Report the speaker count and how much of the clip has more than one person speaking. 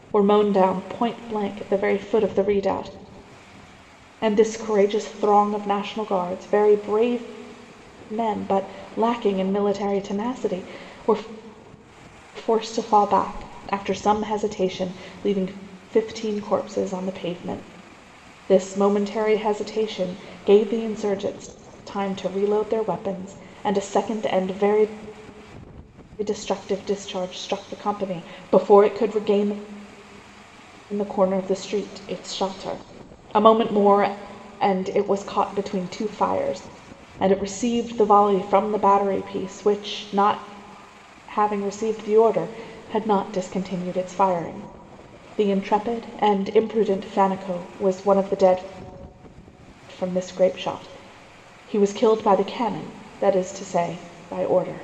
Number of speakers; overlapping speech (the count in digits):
1, no overlap